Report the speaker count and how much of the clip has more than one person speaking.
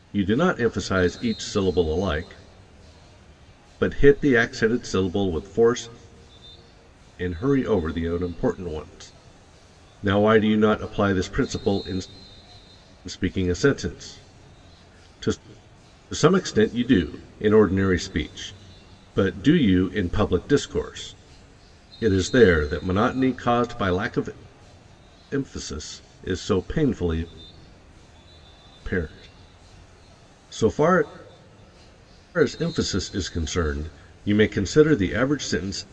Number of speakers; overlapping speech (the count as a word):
one, no overlap